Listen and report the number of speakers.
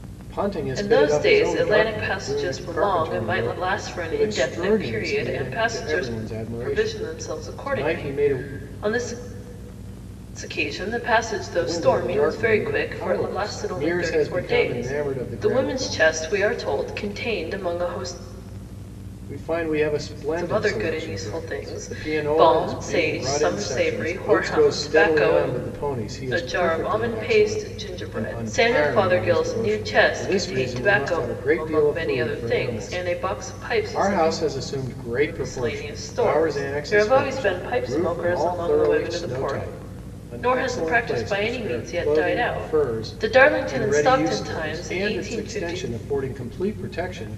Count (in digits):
2